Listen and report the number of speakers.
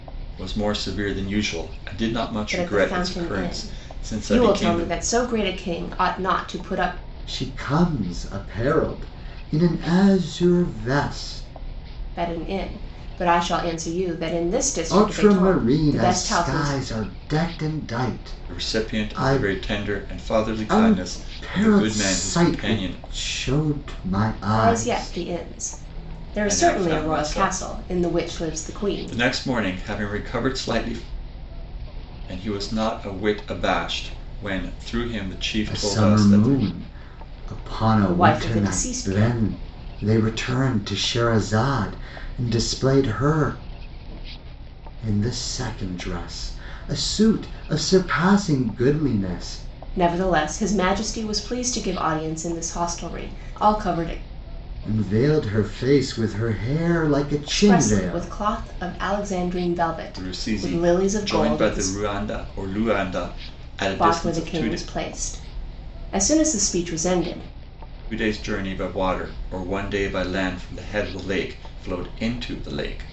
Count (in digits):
3